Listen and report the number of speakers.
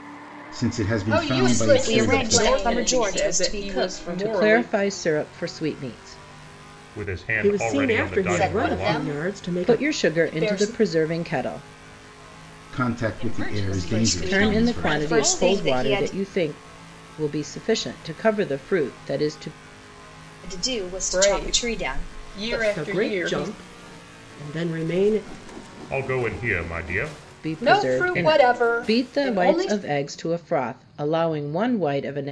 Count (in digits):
8